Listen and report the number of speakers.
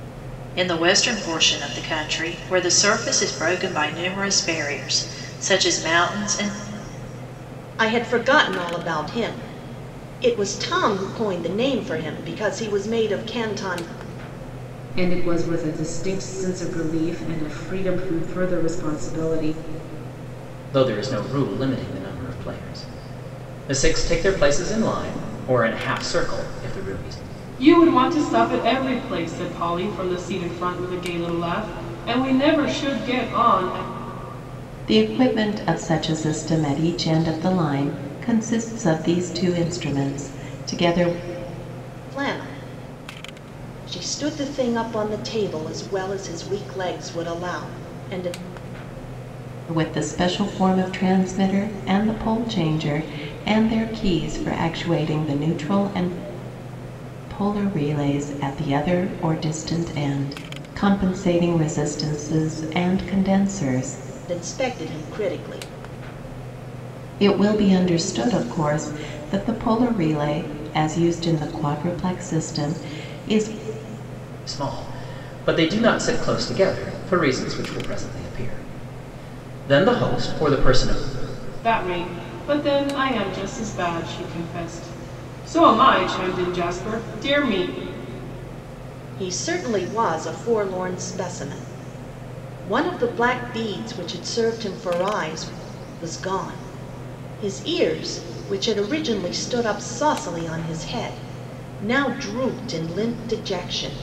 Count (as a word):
six